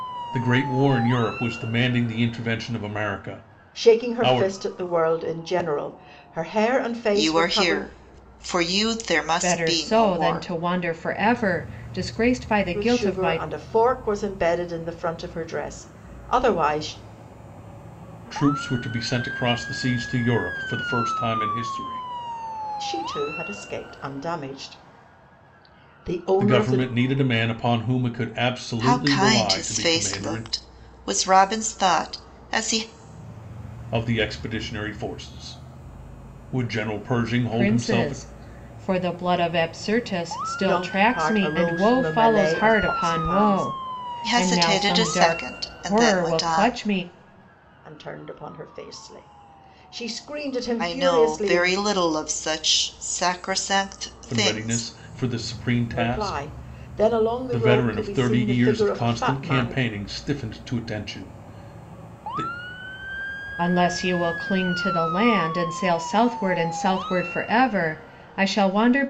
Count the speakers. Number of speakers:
4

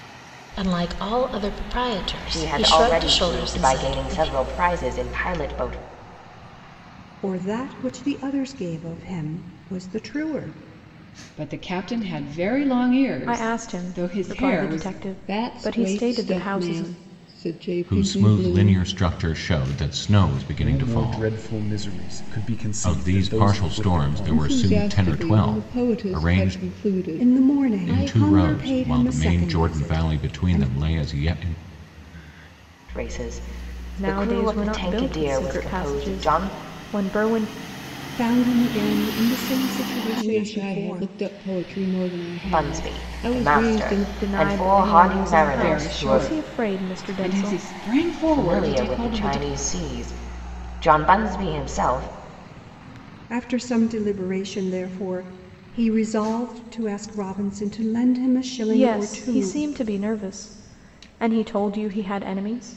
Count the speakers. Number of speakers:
8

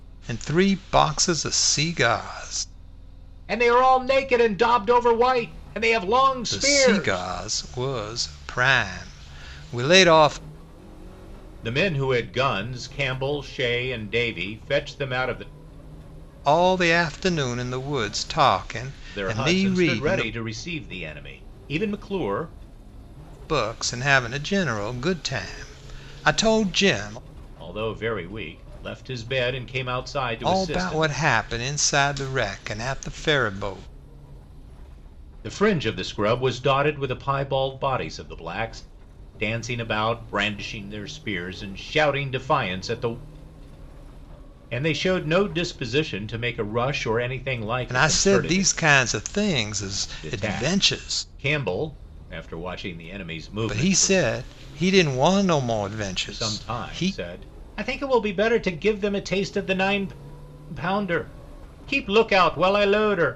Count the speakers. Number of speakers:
2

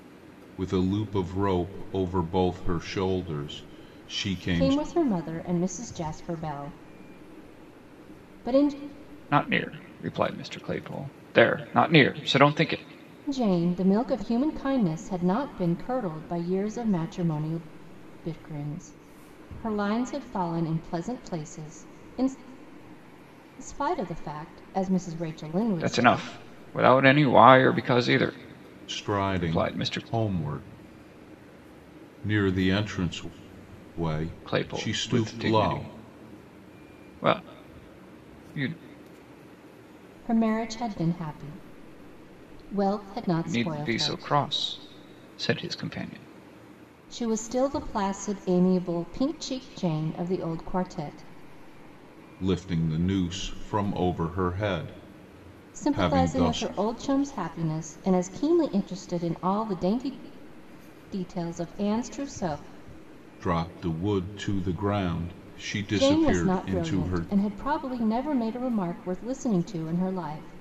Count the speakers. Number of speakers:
3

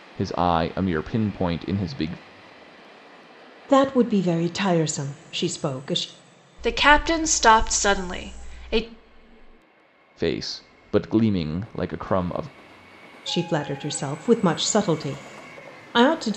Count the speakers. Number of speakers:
3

